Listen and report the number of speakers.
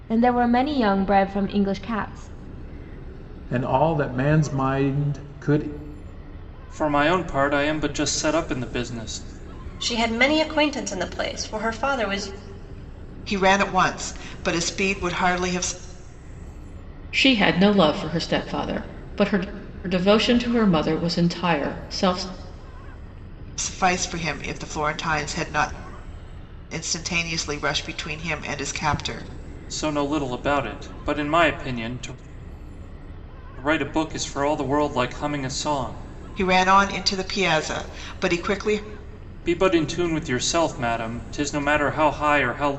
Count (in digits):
6